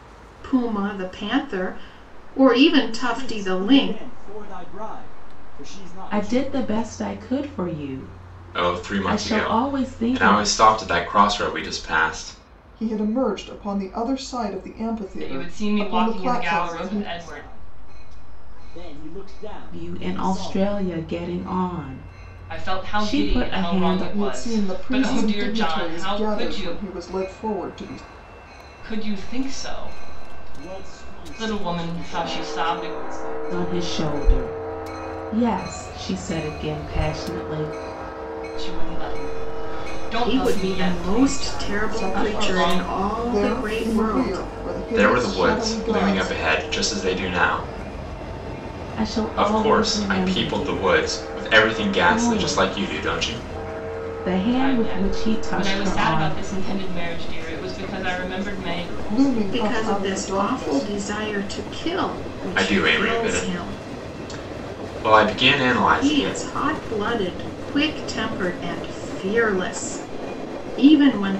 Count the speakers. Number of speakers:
6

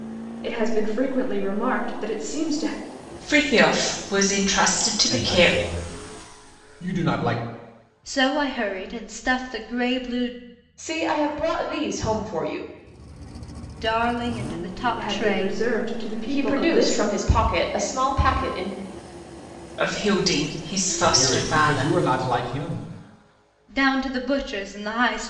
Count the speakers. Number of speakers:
5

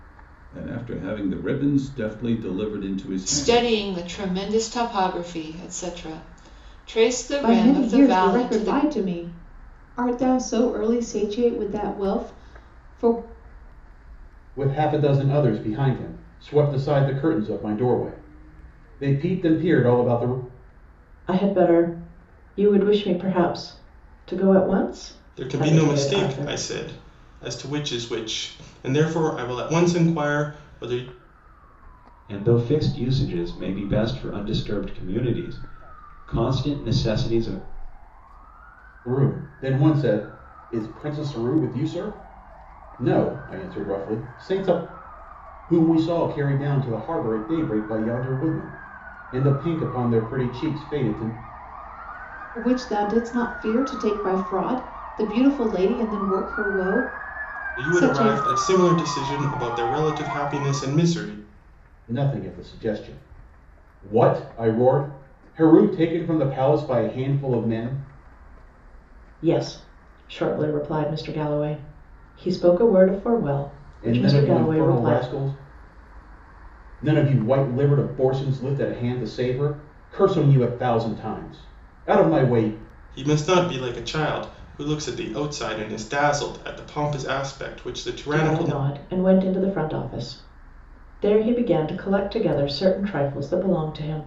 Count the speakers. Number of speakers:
7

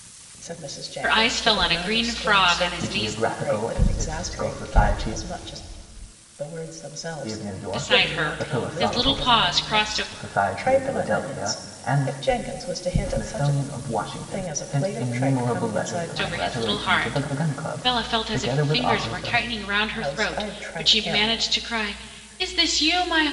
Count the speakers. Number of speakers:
3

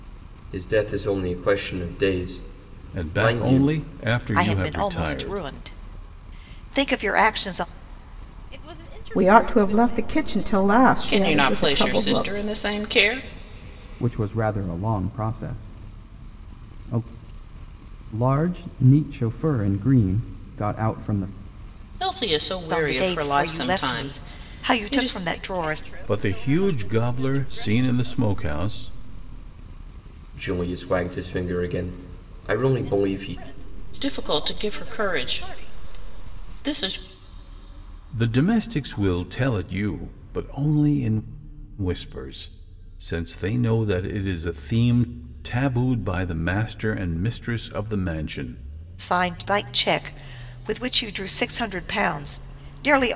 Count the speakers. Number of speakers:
7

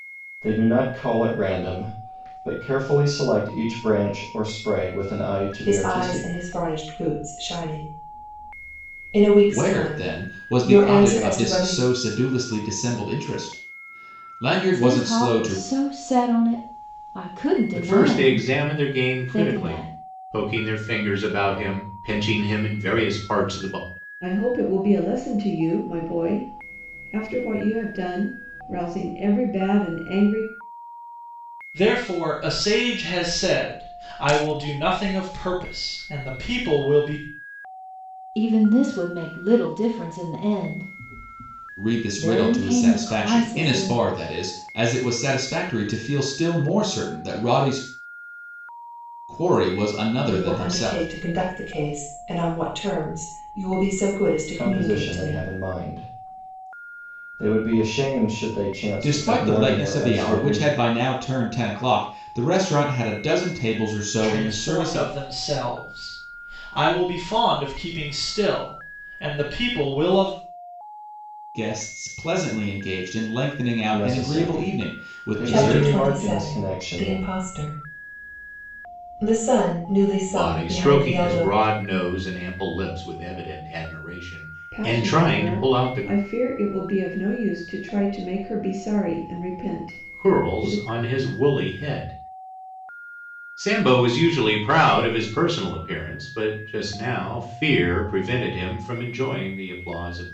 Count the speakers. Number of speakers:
7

